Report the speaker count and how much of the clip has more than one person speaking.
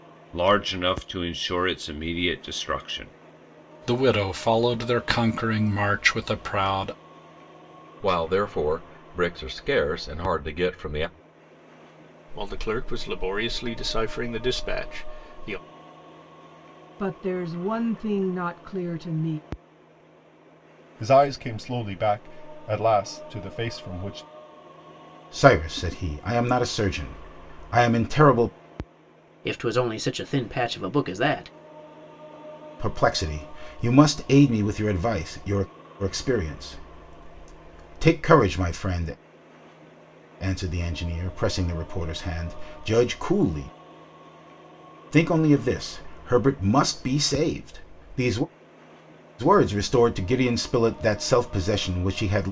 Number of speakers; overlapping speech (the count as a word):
eight, no overlap